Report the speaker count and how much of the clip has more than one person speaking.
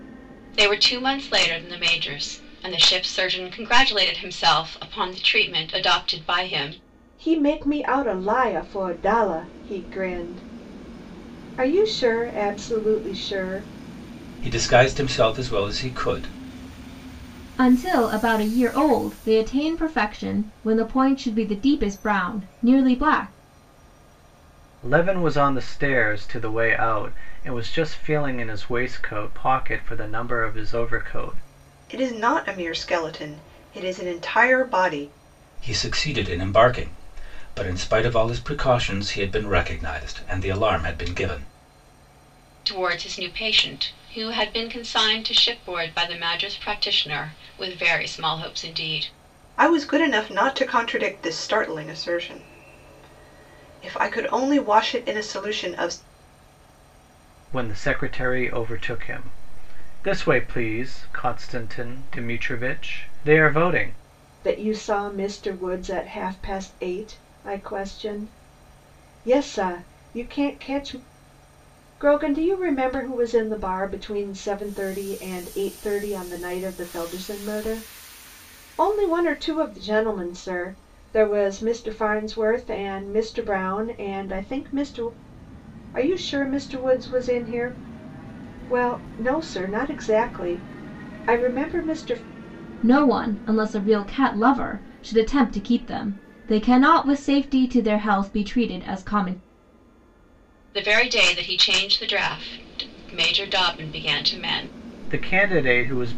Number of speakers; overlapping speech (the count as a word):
six, no overlap